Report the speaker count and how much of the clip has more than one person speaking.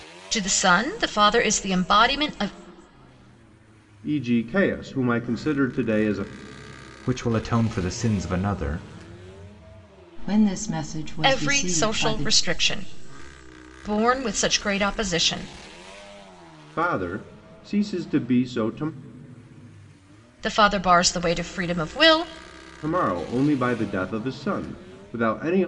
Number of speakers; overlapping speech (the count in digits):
4, about 4%